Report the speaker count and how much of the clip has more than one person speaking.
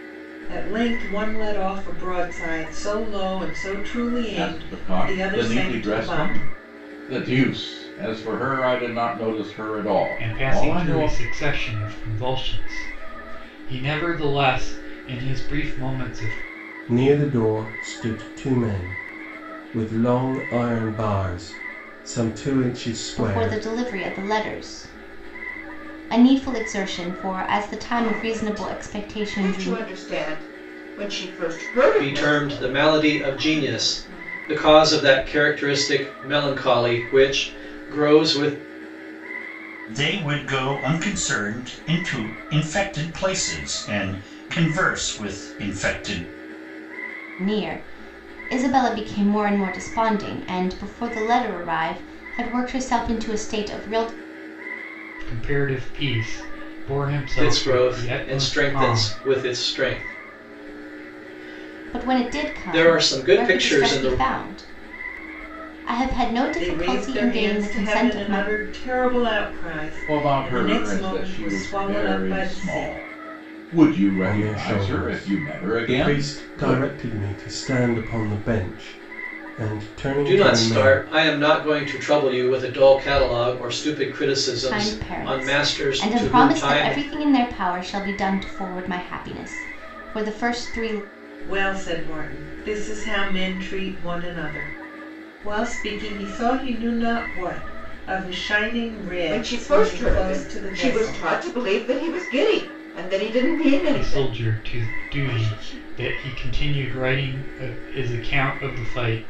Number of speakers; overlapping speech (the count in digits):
8, about 25%